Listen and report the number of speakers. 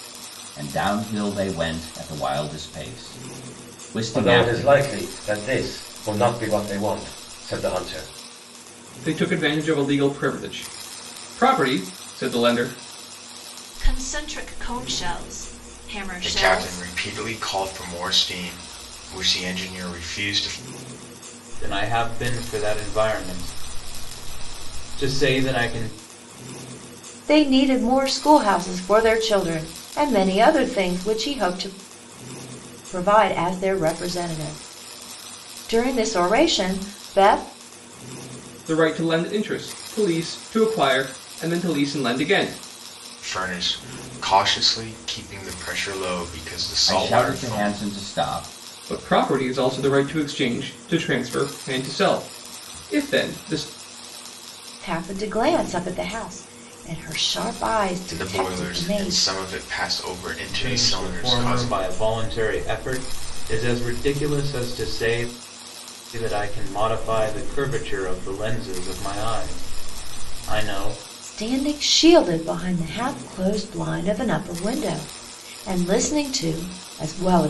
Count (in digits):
7